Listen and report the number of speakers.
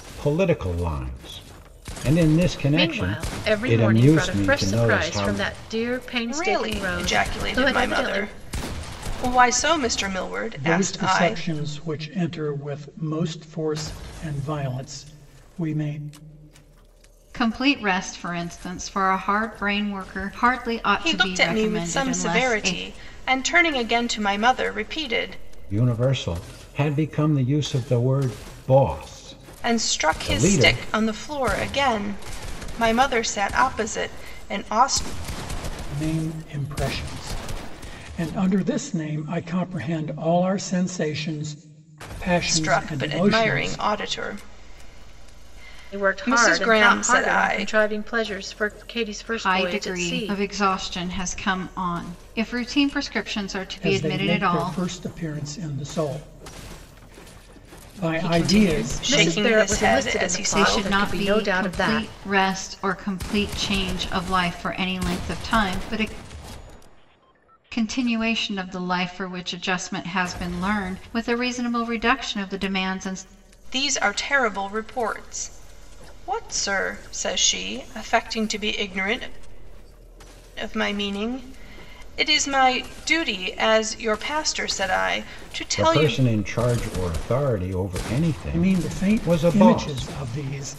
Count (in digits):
5